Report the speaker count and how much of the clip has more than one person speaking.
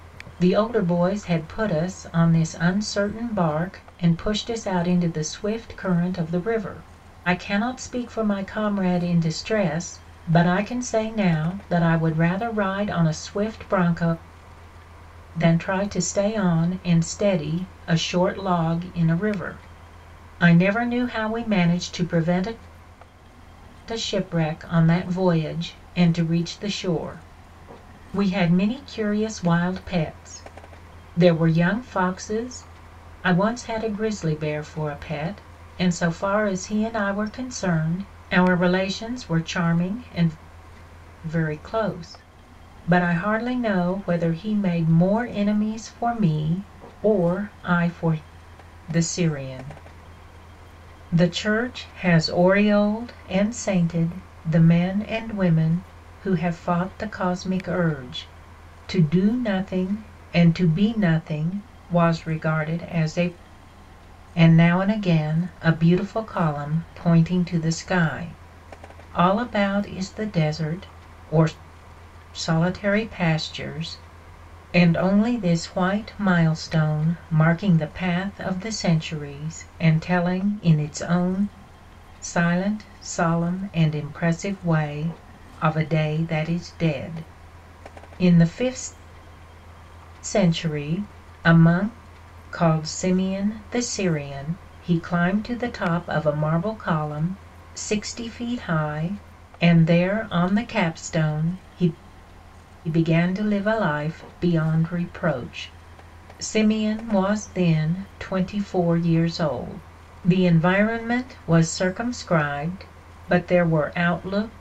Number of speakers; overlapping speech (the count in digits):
1, no overlap